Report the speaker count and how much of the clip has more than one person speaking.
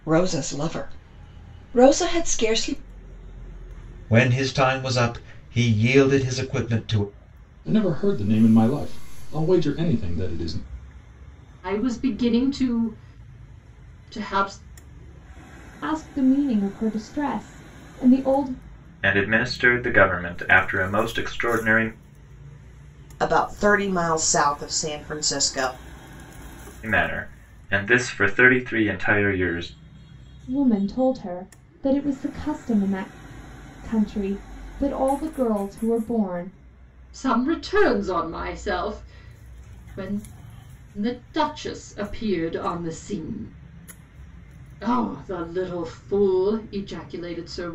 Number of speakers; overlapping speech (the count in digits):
7, no overlap